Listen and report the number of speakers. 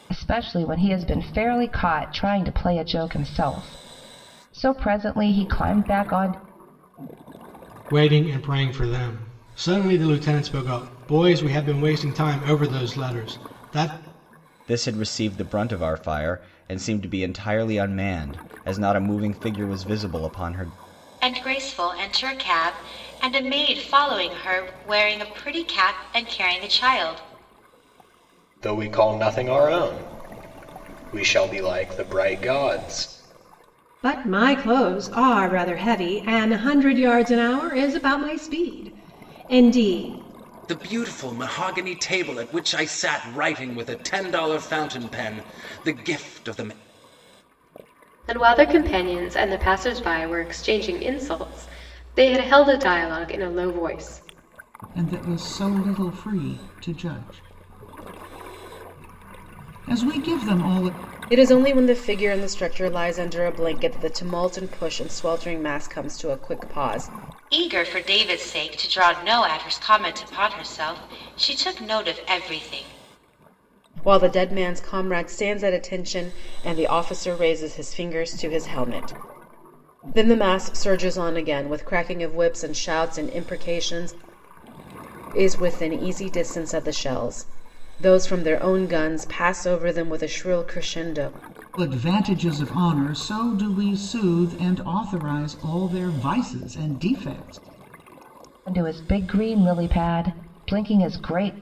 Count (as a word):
ten